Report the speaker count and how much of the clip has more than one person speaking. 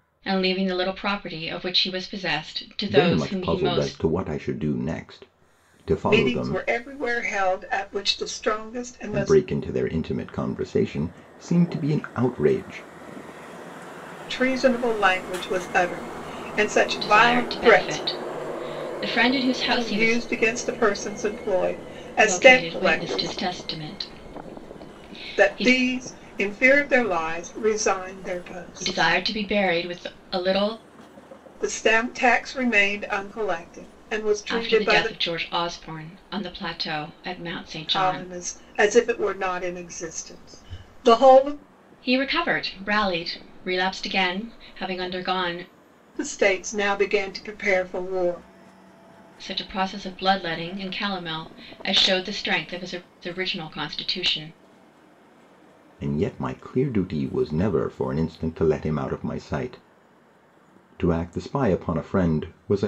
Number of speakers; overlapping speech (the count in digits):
3, about 11%